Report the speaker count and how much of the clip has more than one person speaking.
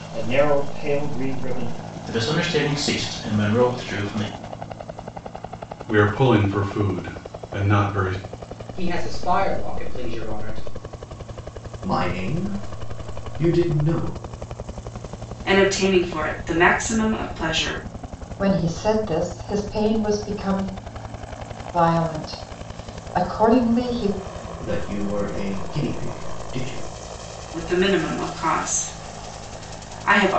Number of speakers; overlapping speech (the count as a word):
seven, no overlap